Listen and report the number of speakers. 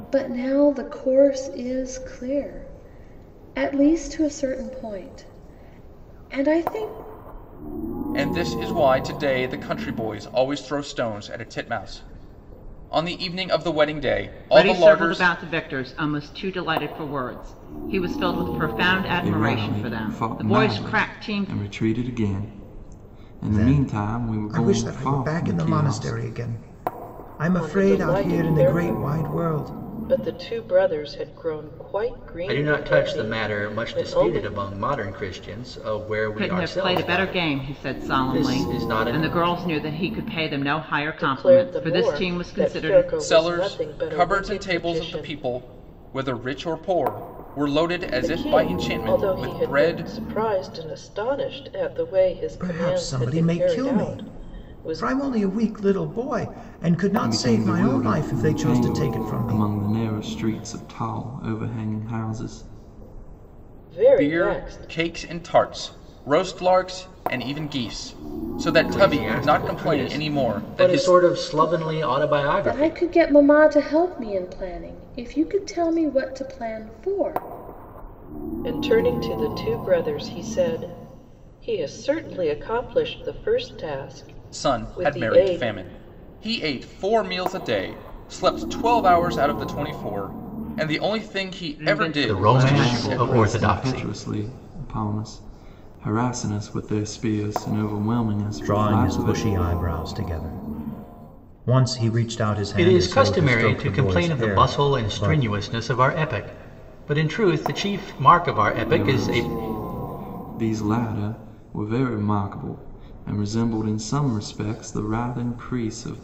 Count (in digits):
7